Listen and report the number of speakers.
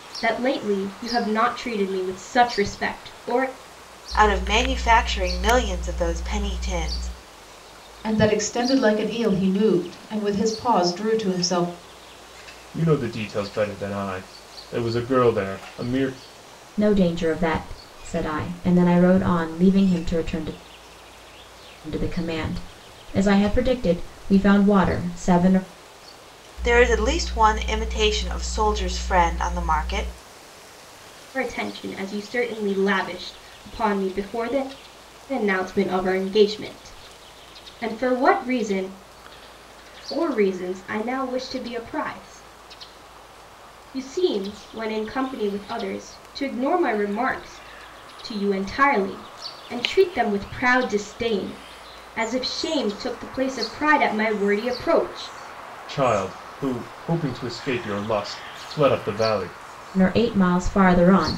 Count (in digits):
5